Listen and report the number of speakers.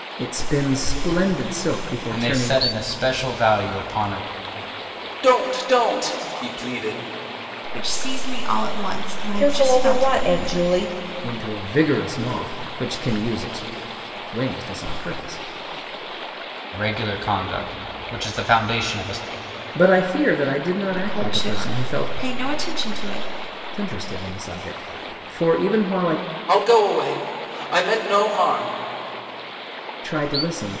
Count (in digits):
5